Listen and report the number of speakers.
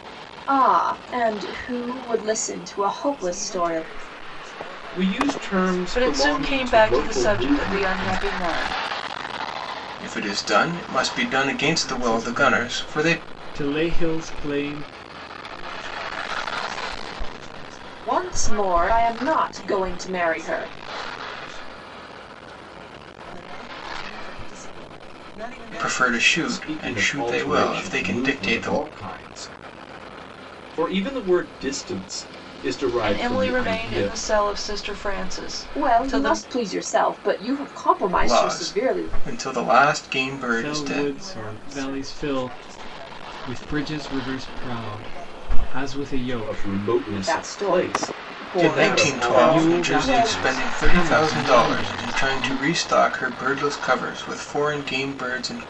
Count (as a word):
six